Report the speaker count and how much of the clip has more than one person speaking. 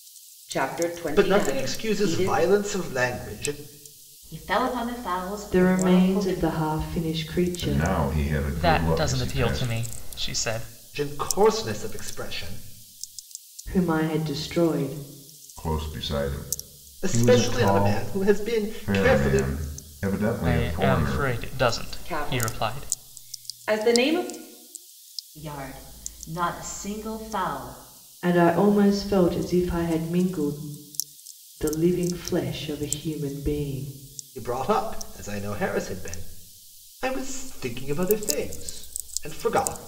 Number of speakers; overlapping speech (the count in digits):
6, about 19%